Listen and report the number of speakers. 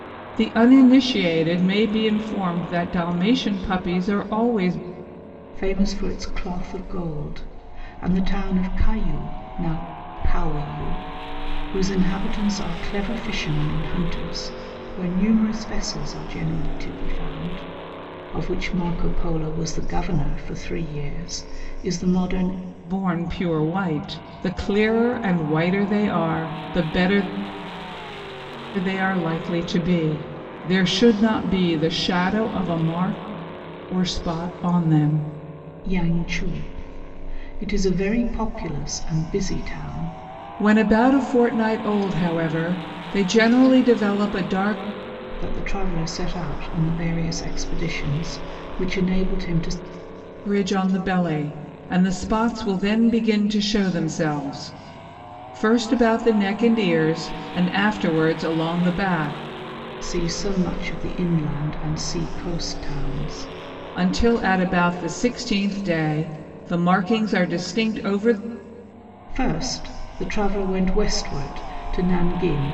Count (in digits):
2